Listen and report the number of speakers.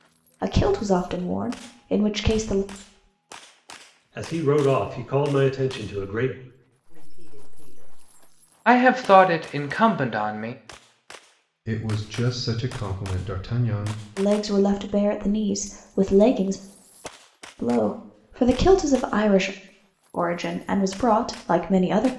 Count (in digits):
5